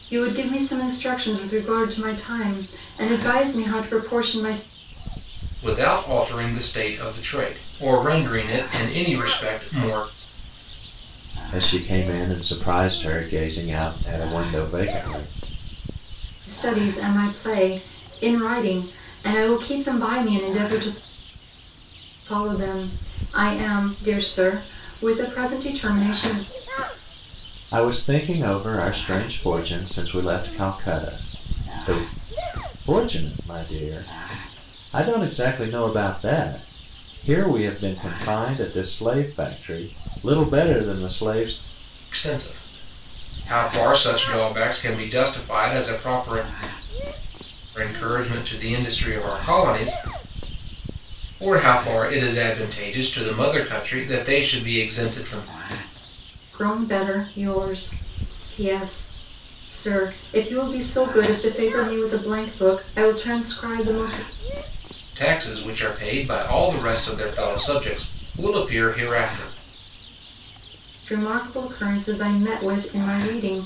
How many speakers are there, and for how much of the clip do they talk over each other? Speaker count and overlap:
three, no overlap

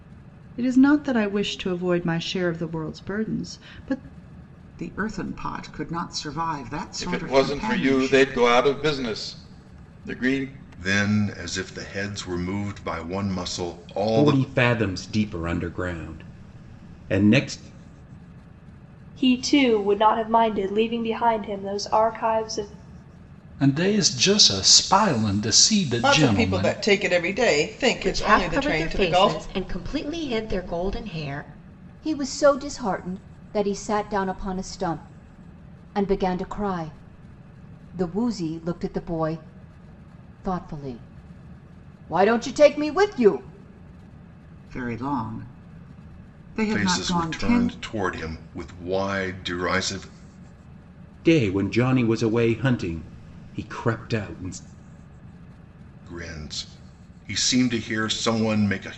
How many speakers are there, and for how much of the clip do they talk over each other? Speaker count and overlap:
ten, about 9%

